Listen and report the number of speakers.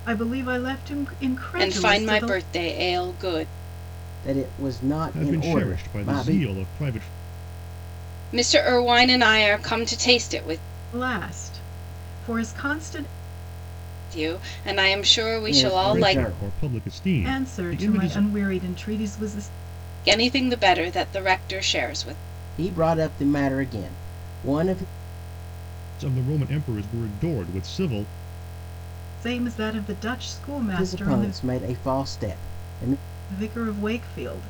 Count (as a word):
four